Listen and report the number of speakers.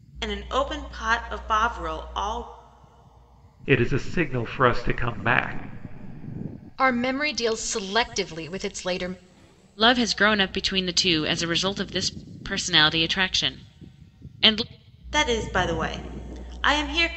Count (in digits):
4